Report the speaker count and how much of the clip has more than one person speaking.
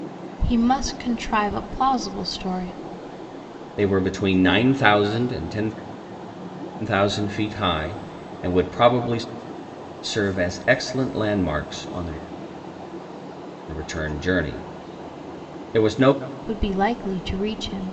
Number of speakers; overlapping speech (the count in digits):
2, no overlap